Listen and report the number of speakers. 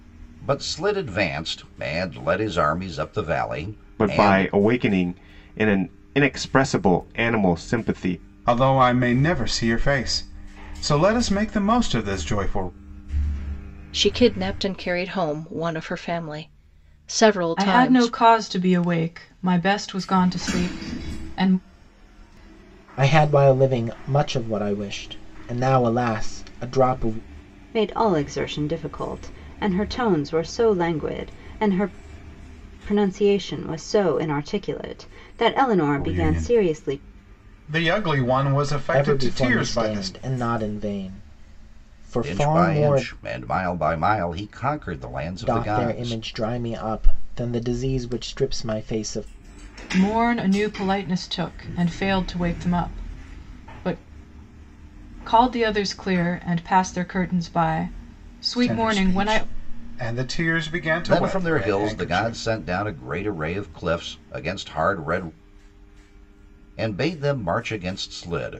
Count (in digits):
7